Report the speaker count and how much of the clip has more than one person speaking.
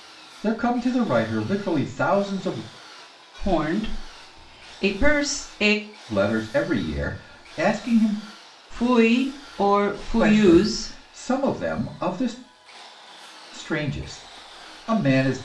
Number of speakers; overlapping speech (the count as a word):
two, about 6%